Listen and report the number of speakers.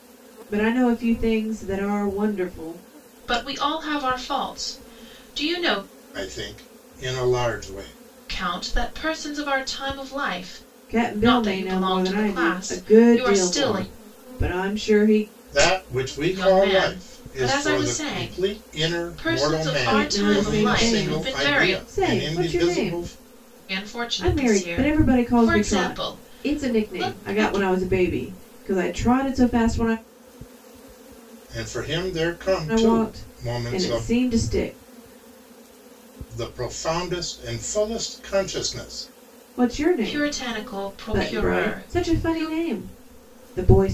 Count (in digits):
3